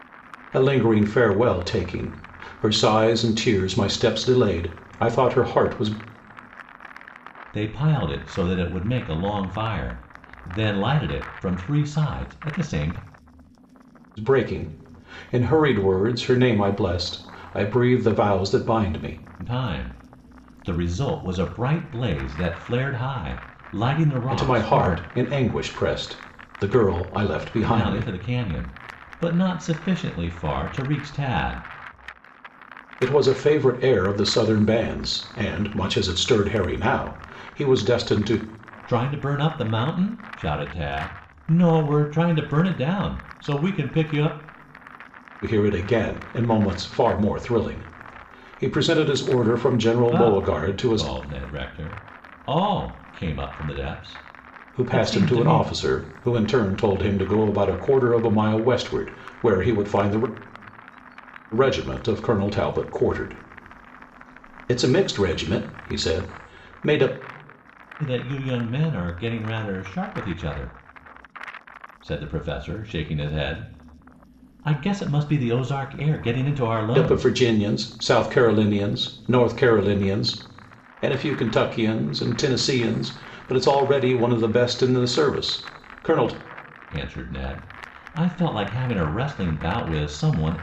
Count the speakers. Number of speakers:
two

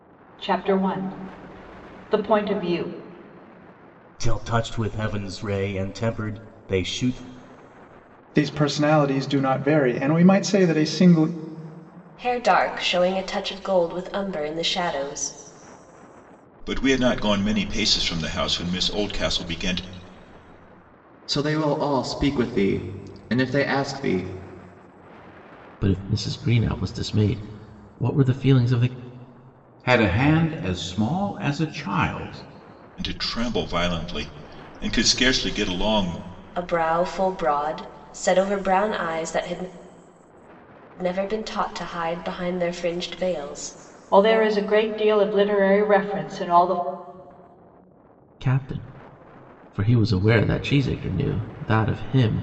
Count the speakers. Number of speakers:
eight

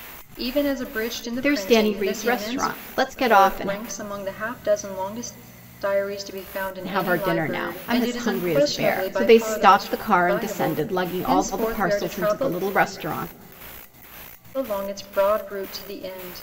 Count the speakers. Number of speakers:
two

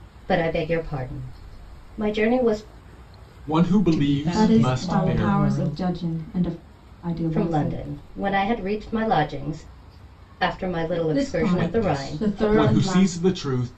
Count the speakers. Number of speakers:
four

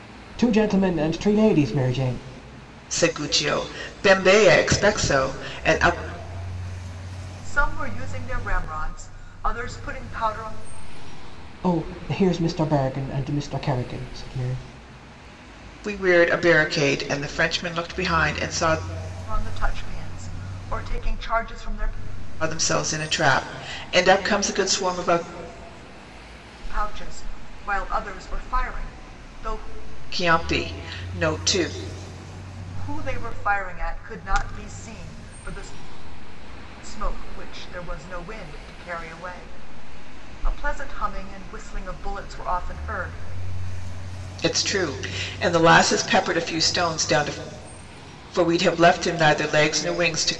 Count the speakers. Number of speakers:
three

